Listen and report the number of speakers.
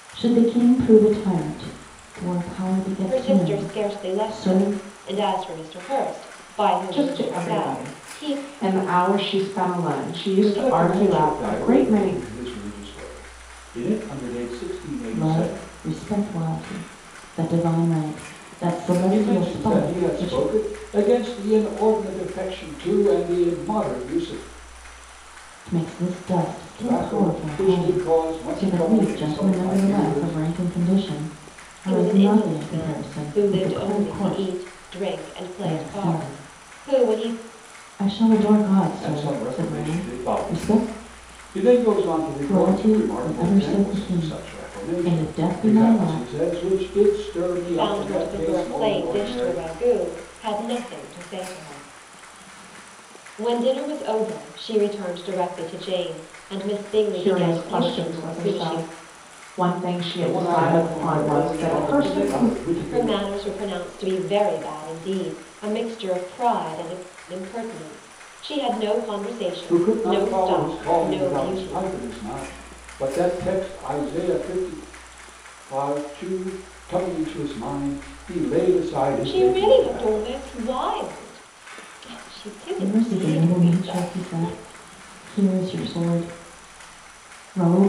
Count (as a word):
four